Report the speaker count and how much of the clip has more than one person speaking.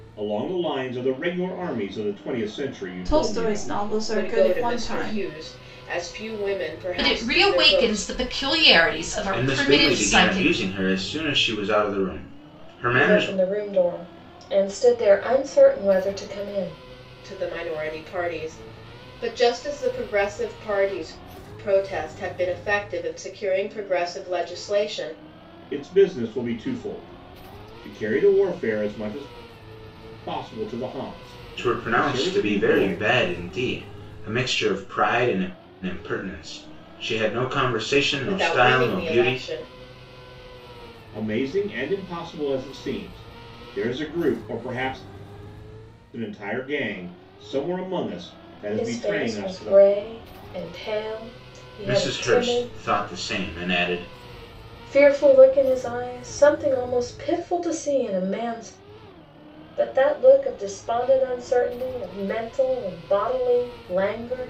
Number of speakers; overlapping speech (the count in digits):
6, about 15%